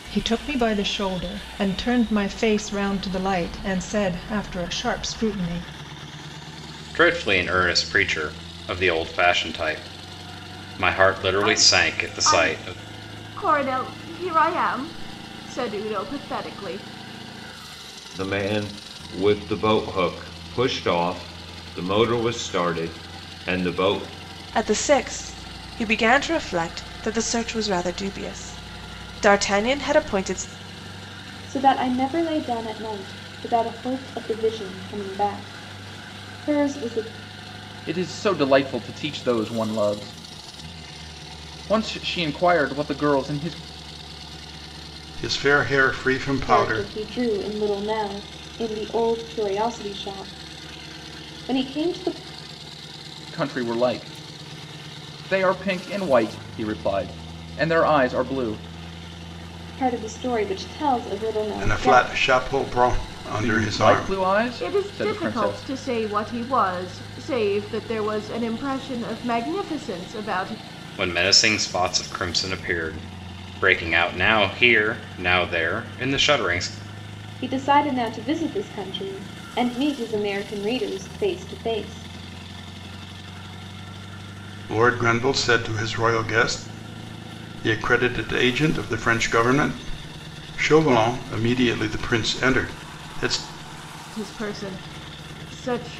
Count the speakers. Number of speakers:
8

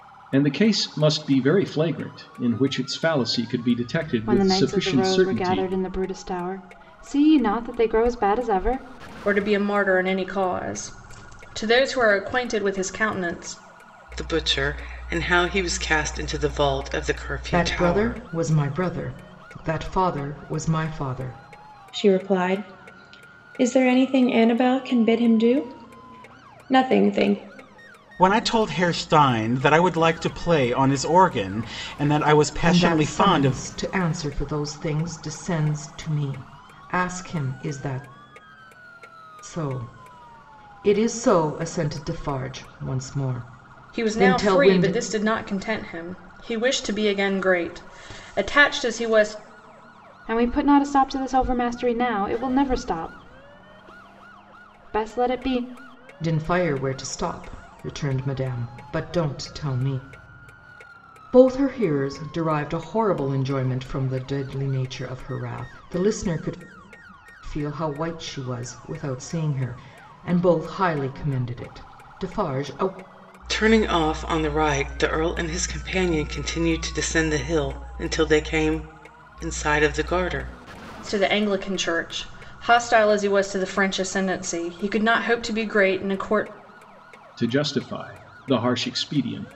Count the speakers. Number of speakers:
7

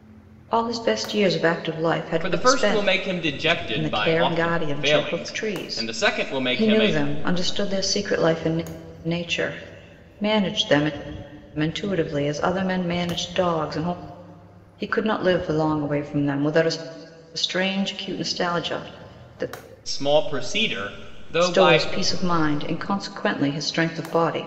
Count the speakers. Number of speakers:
2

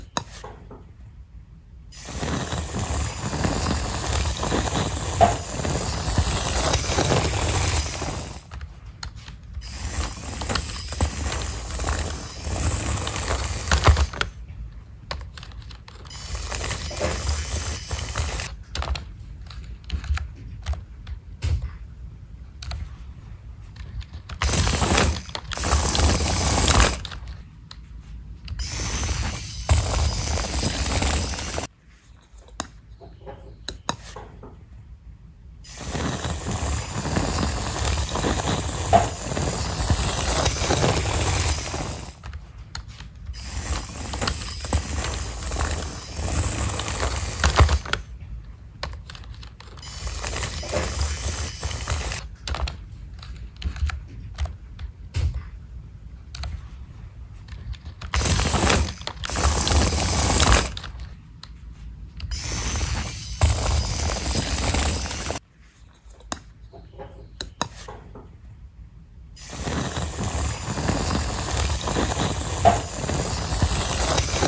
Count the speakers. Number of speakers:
0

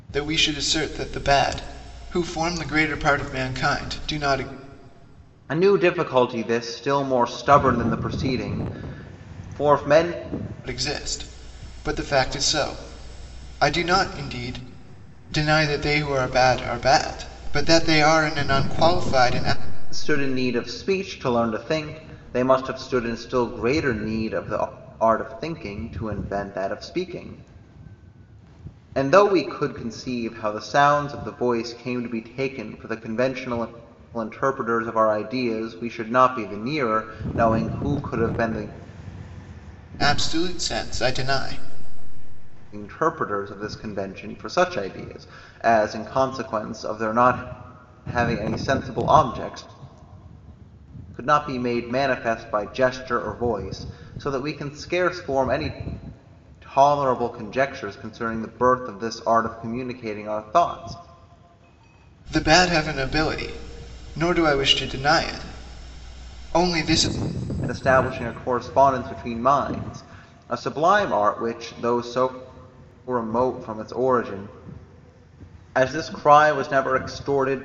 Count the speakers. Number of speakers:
2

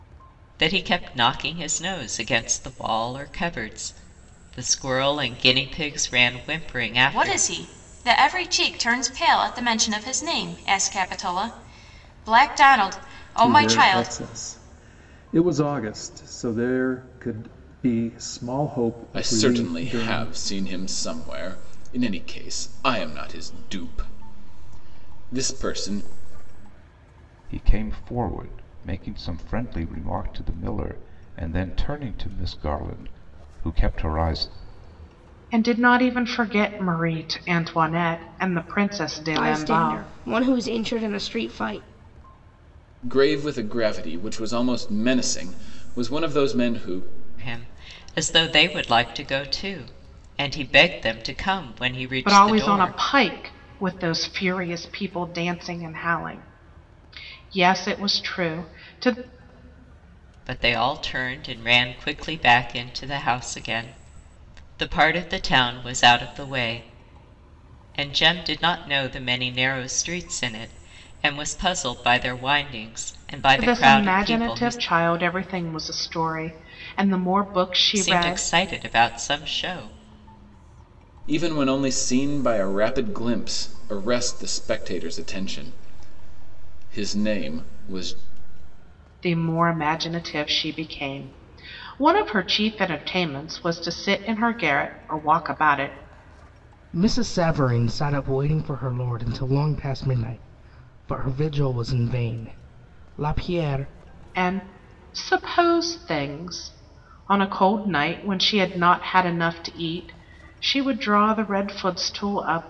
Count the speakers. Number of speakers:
7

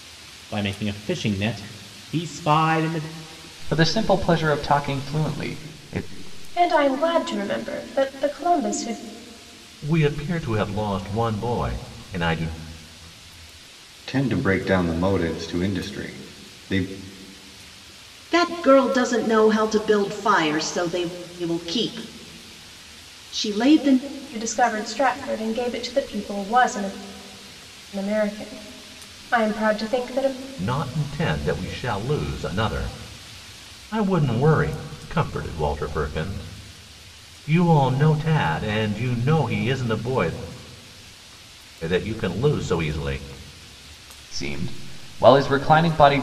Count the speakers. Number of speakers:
6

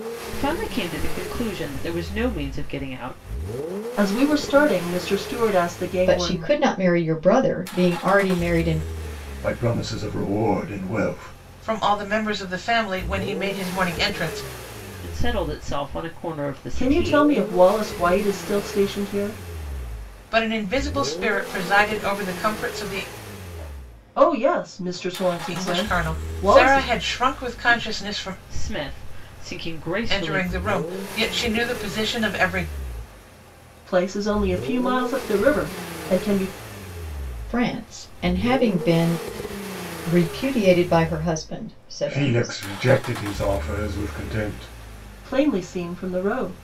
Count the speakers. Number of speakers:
5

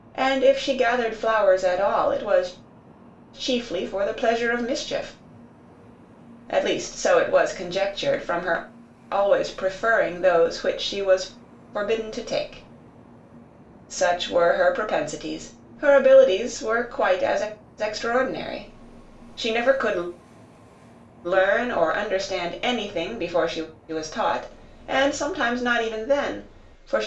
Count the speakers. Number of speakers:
1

